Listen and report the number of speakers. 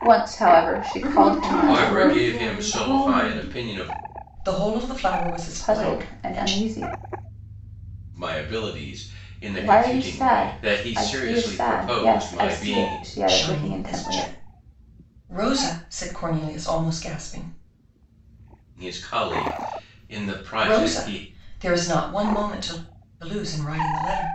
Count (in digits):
4